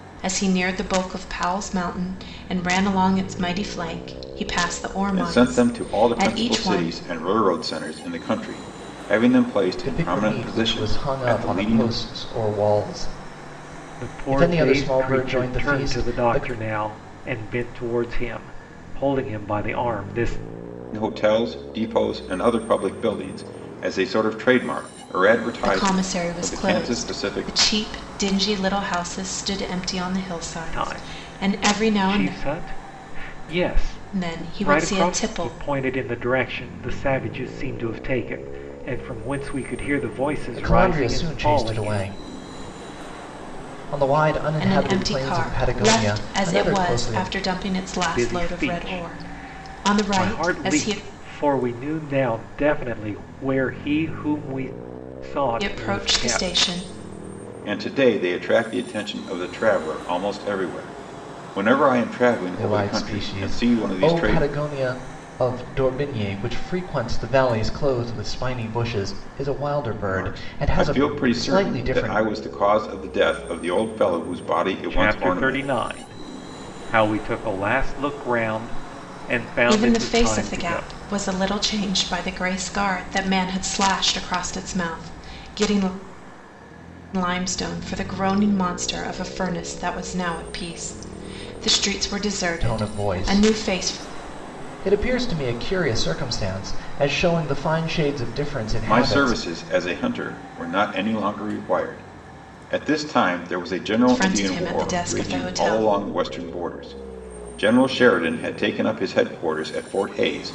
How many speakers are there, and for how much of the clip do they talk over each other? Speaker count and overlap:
four, about 27%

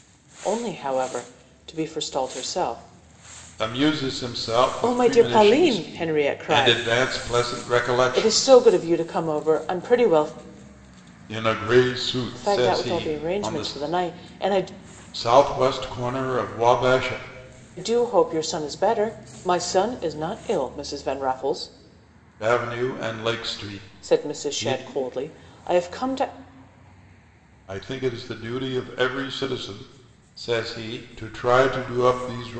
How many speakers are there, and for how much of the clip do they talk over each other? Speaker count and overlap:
two, about 13%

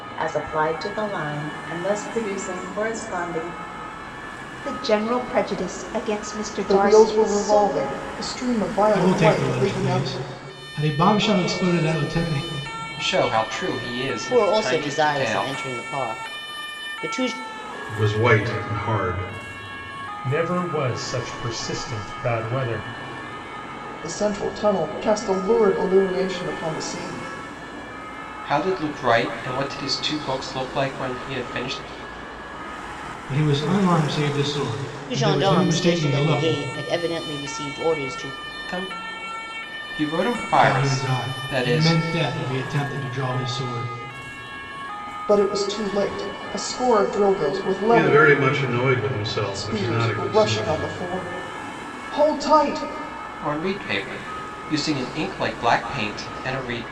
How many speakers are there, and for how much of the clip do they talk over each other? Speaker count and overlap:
eight, about 15%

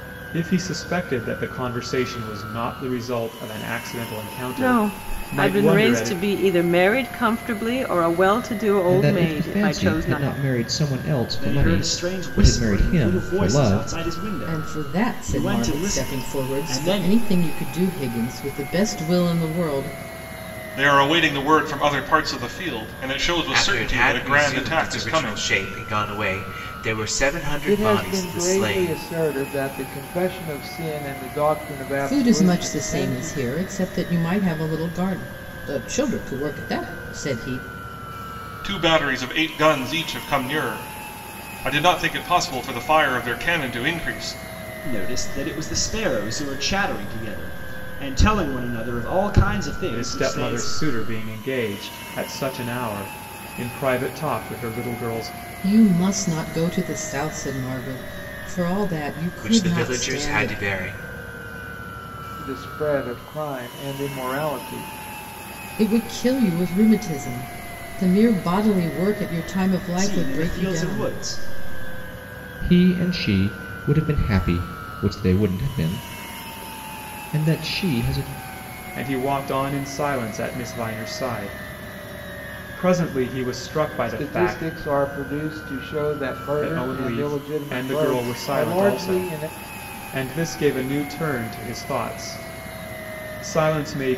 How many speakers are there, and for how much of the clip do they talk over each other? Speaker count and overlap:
eight, about 21%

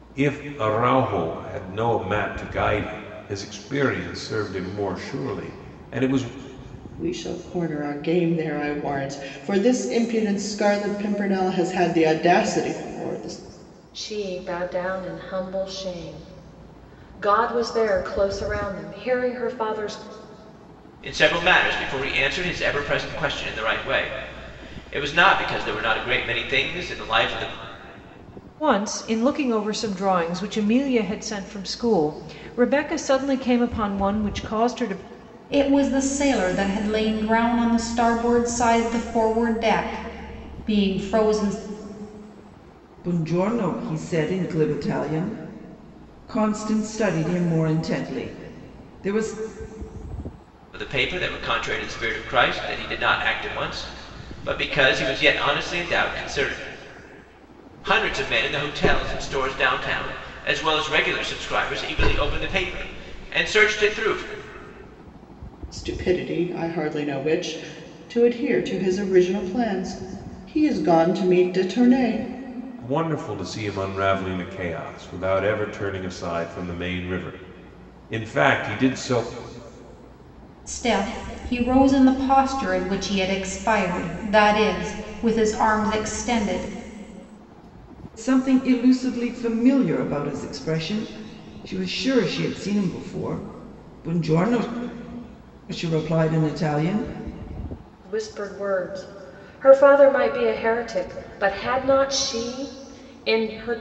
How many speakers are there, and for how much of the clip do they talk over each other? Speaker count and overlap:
seven, no overlap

